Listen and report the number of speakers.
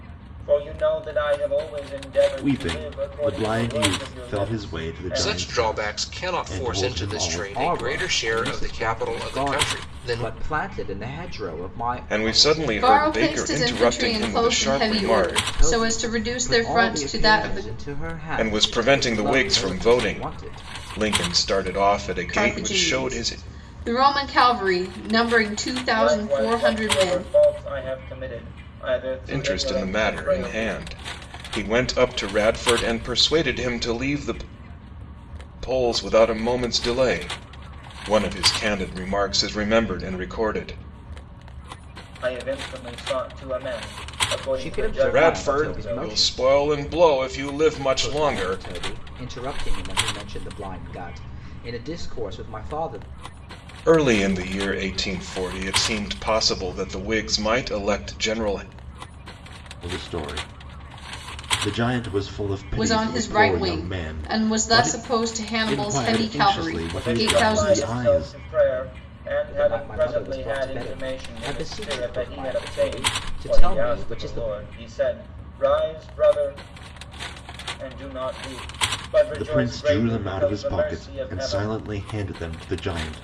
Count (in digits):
6